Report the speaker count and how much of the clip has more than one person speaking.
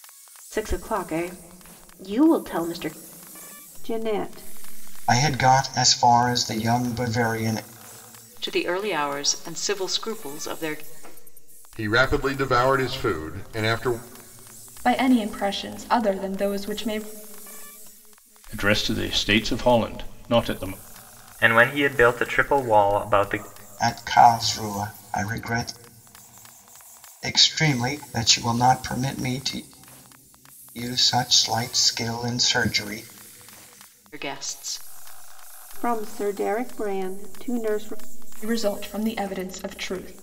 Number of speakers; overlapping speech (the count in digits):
8, no overlap